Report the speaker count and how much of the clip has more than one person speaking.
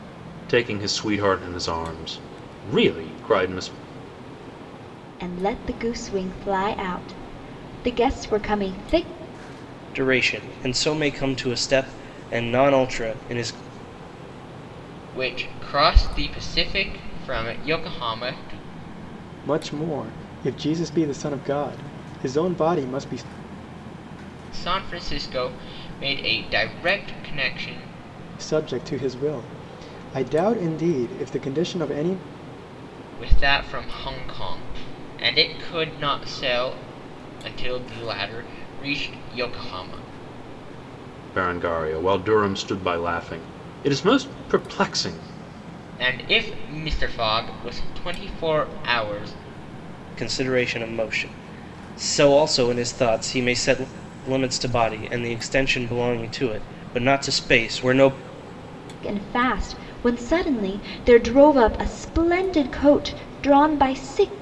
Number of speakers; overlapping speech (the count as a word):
five, no overlap